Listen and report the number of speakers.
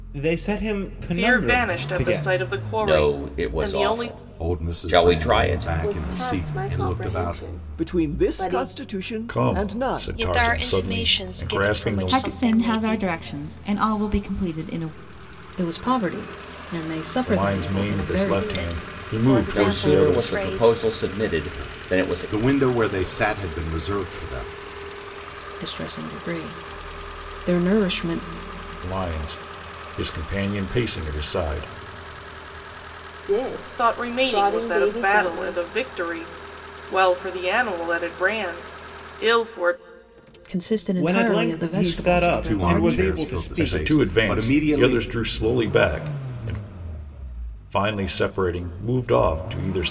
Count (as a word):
ten